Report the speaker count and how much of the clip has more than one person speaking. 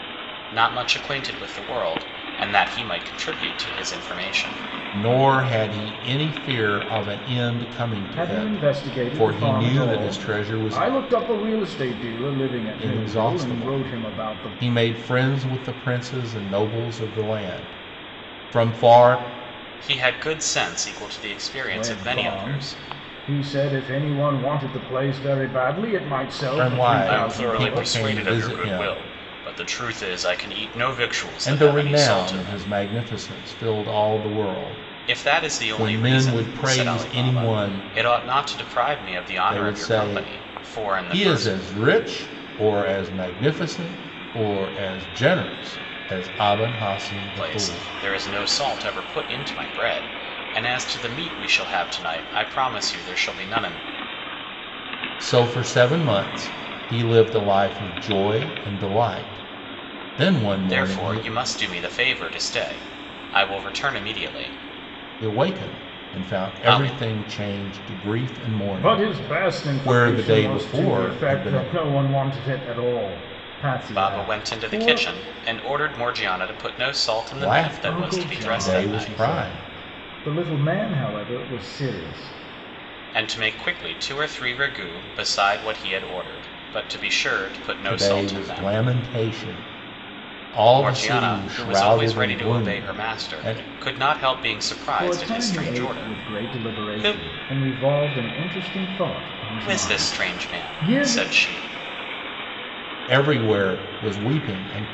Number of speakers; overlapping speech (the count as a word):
three, about 30%